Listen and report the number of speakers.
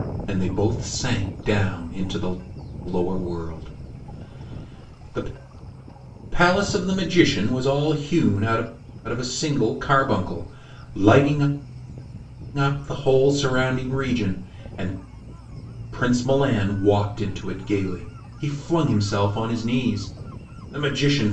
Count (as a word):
one